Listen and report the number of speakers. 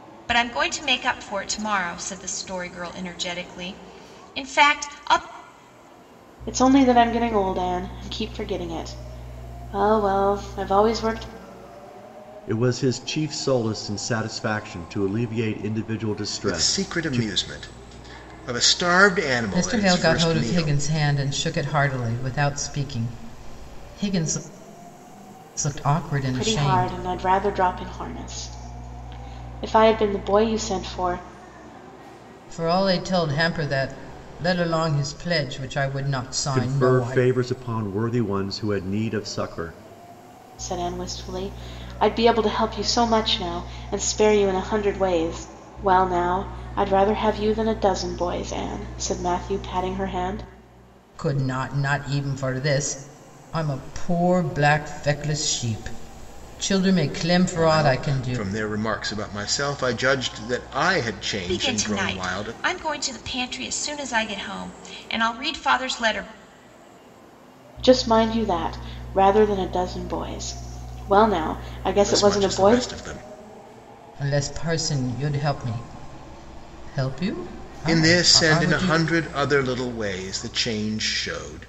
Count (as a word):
five